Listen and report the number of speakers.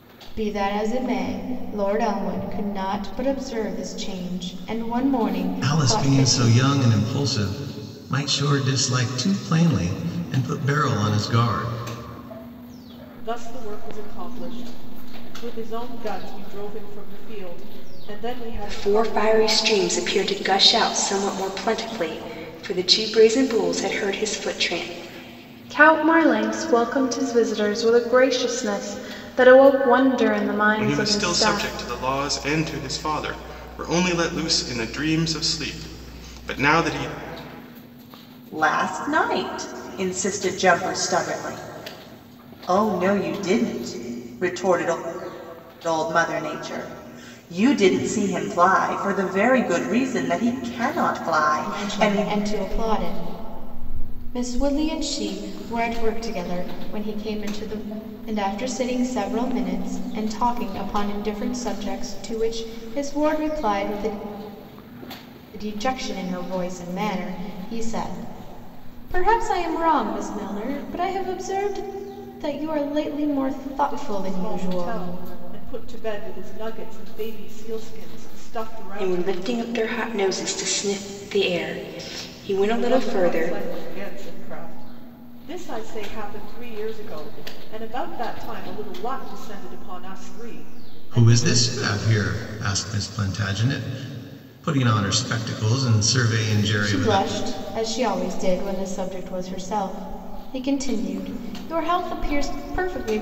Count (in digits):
7